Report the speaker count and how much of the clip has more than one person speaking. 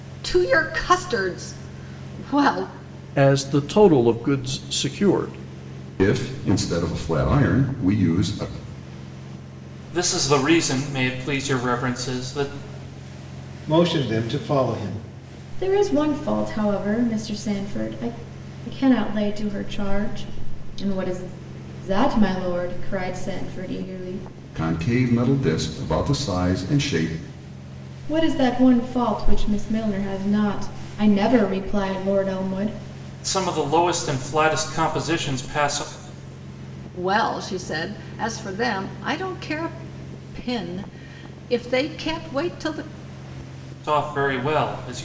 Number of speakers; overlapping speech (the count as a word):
six, no overlap